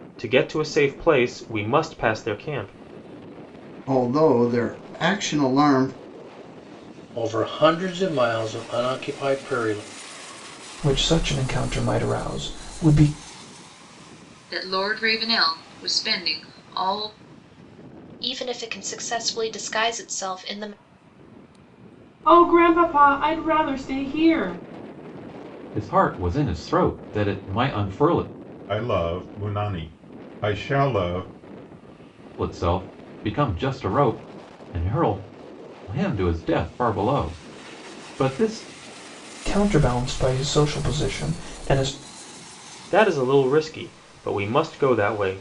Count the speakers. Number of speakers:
9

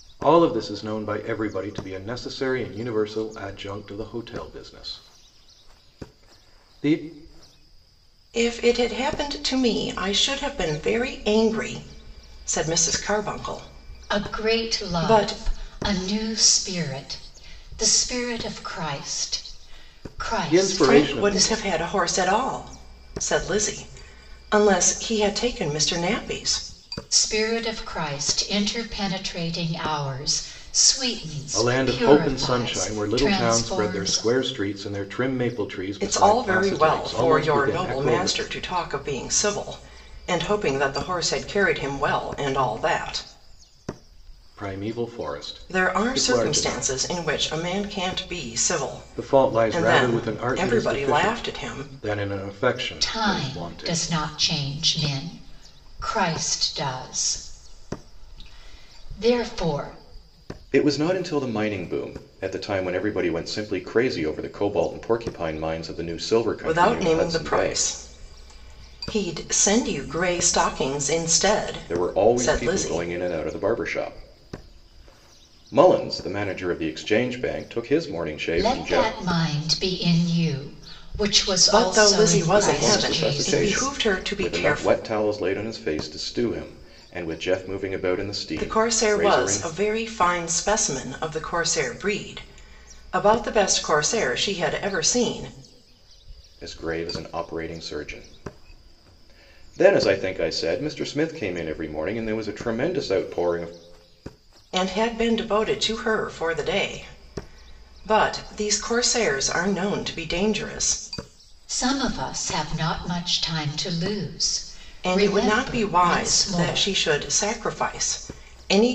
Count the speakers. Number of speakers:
3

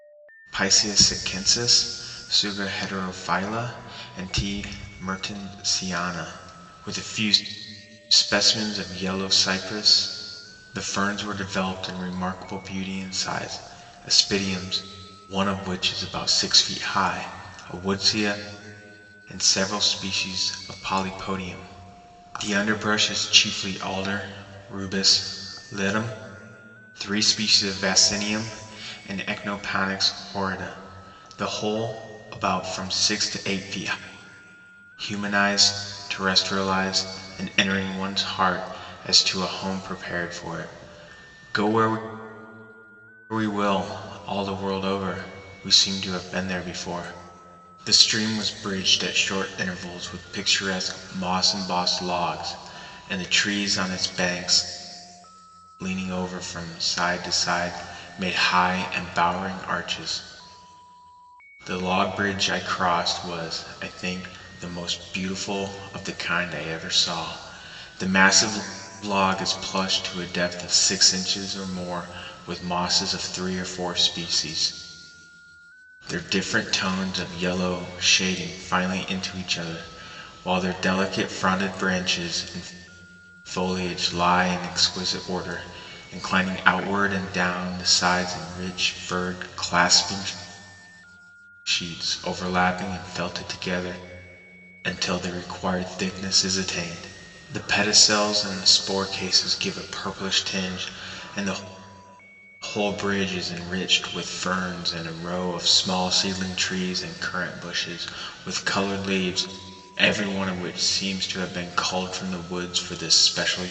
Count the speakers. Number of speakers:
1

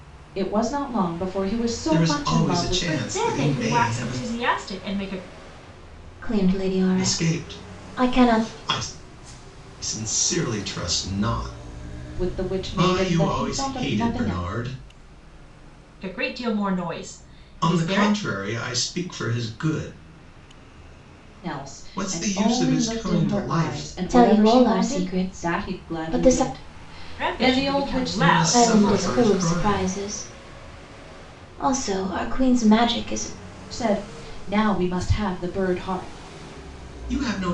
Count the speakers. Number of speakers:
4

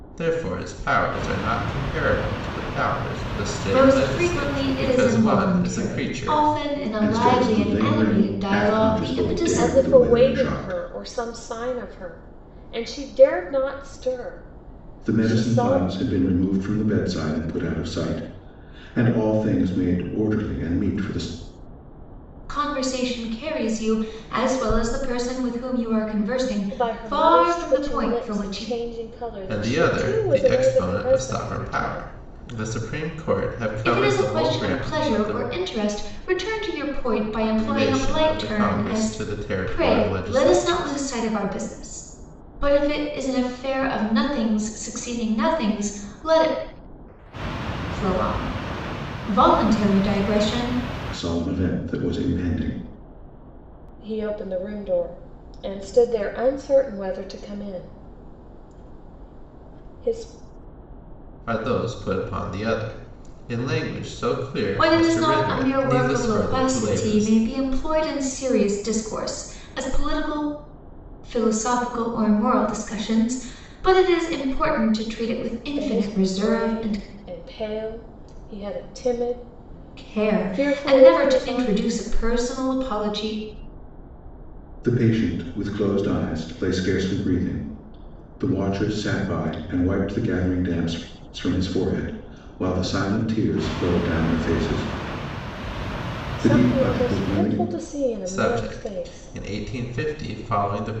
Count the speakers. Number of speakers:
4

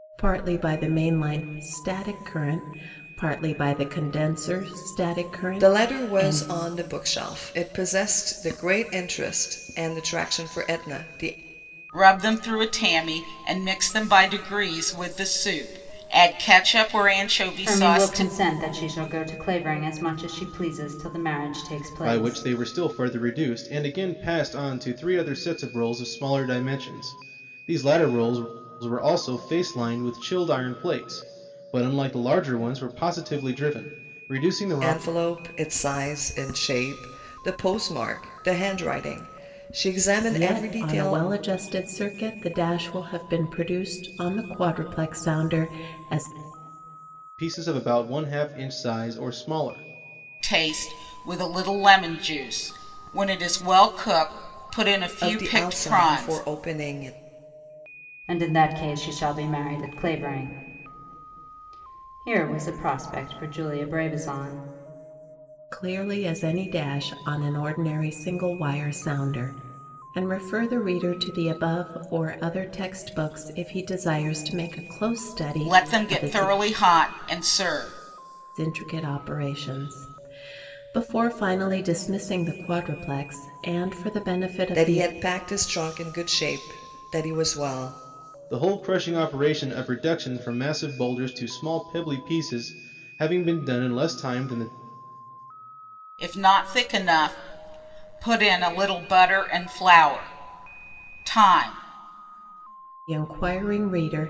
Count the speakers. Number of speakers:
5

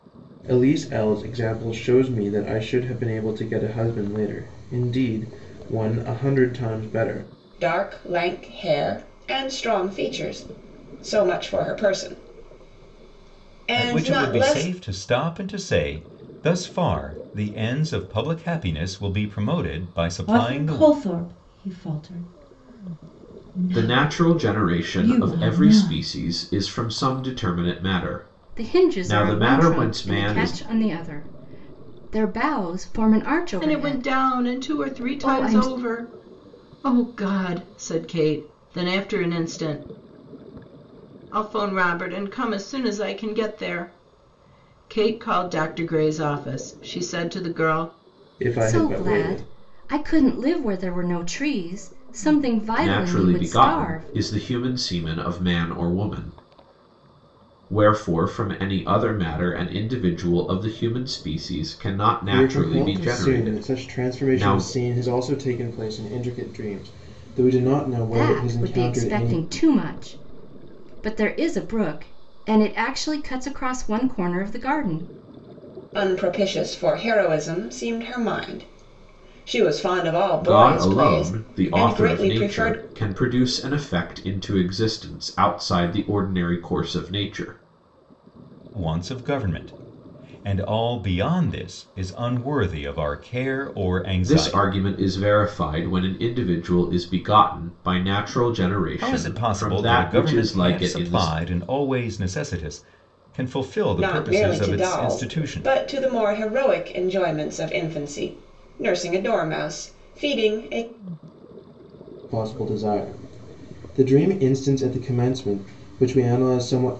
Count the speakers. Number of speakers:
7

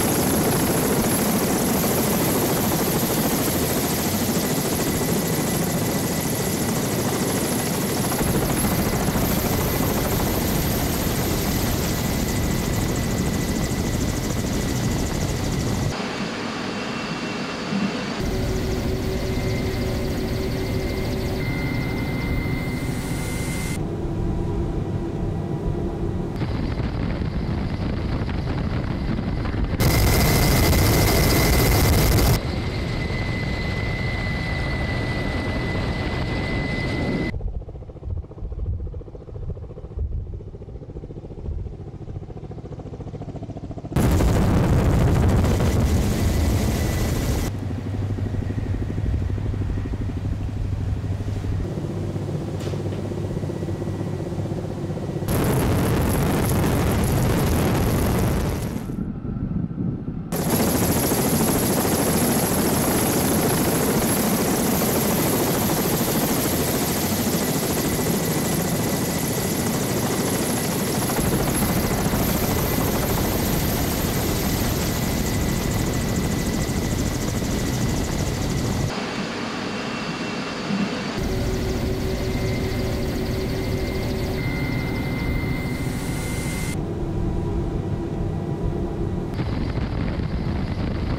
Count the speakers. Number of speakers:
0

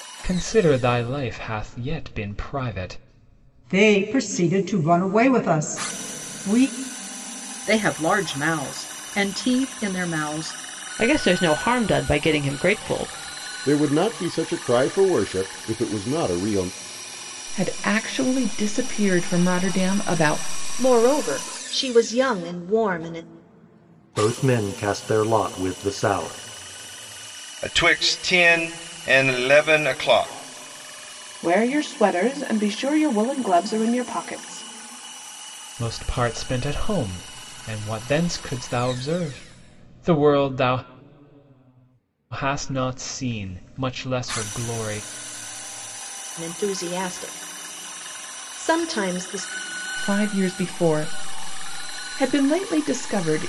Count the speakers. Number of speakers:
10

